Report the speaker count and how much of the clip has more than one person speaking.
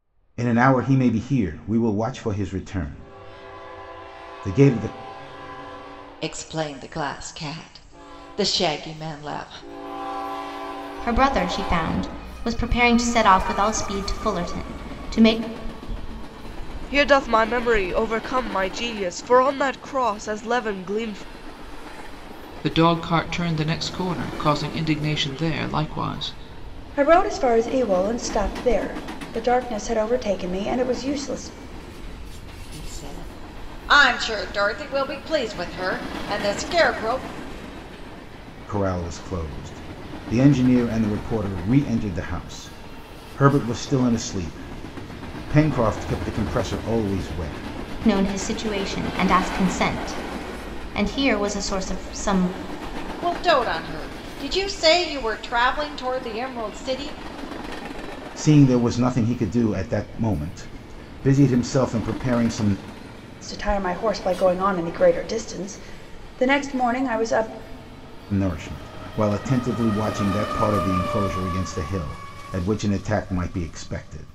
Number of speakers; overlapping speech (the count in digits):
6, no overlap